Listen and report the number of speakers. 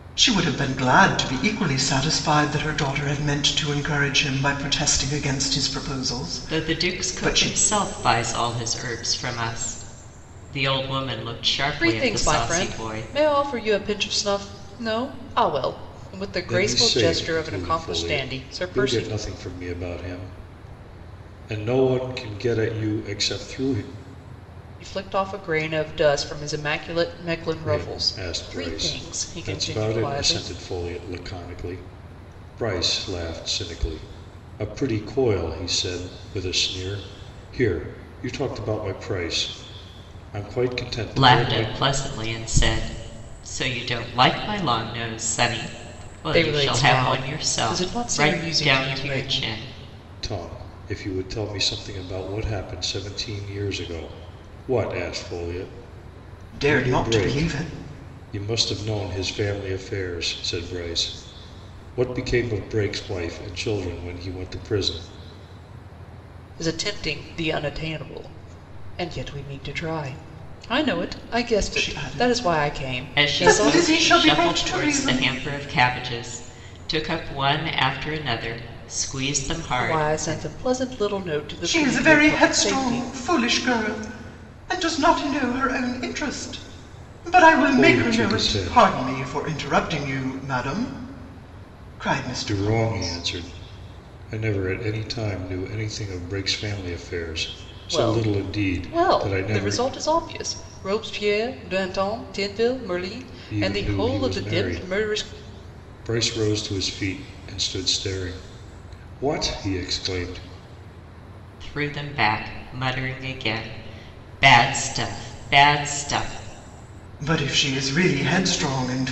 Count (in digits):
4